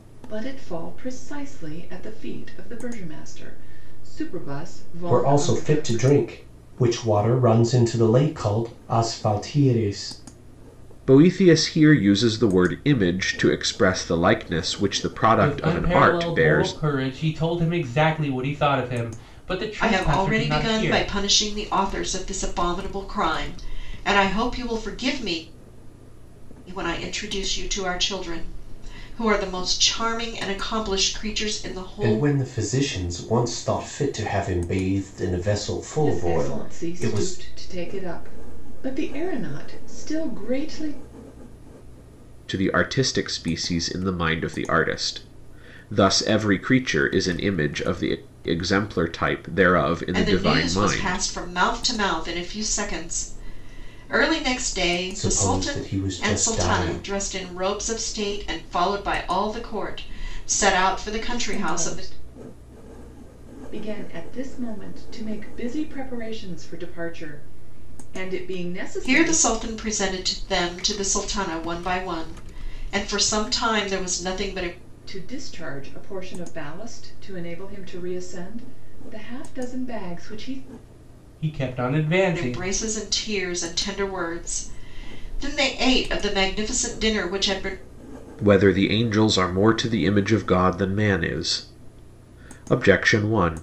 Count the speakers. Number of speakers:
5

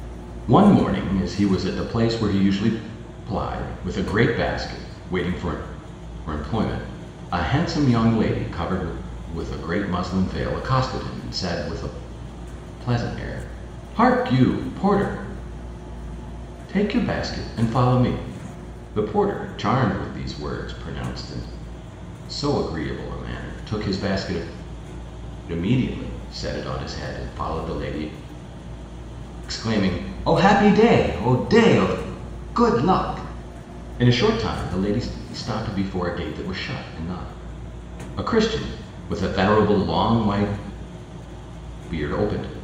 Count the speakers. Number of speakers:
1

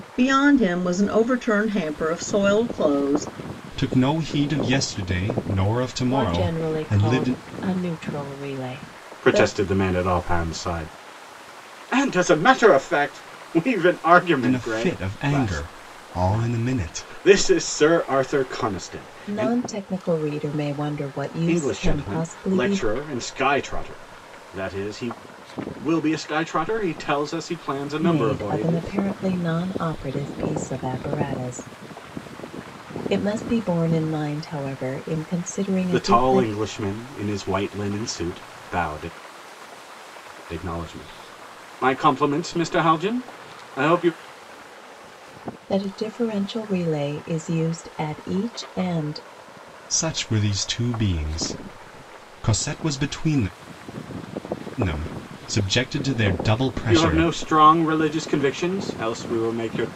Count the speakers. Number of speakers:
4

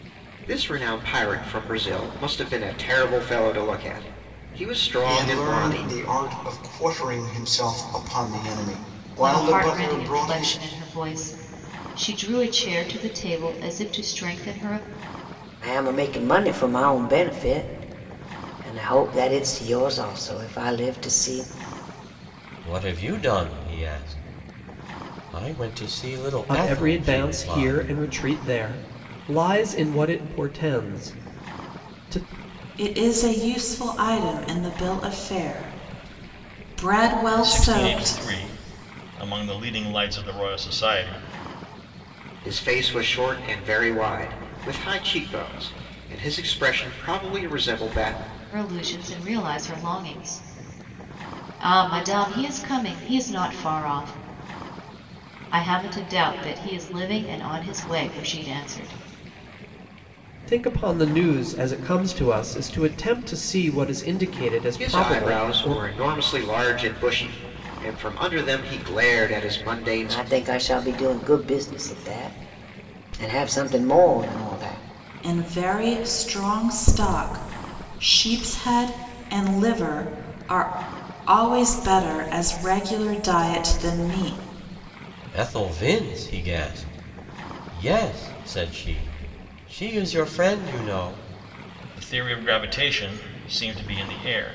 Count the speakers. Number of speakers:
8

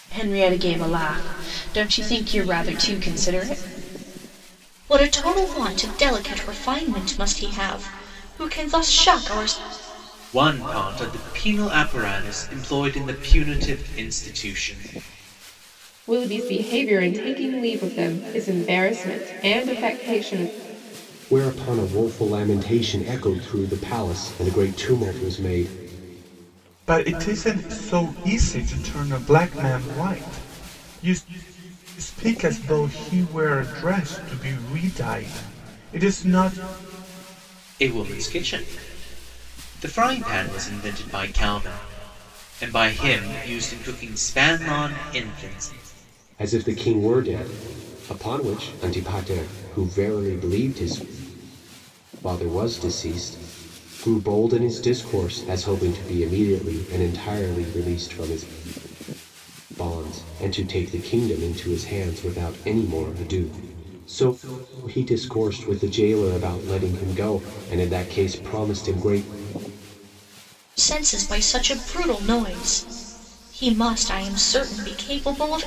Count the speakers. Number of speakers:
6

